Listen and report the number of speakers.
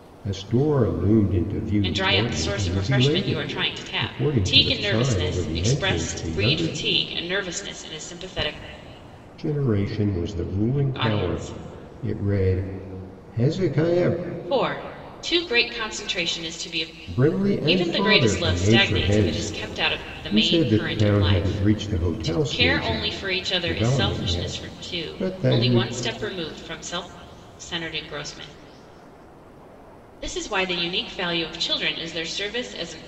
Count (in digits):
2